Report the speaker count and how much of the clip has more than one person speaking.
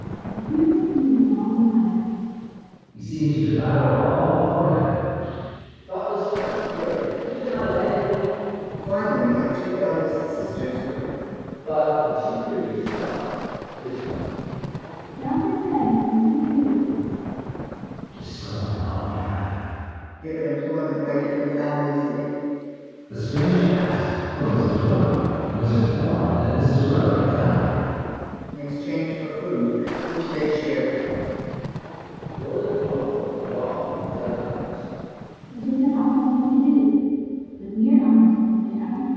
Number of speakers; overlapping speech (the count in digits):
4, no overlap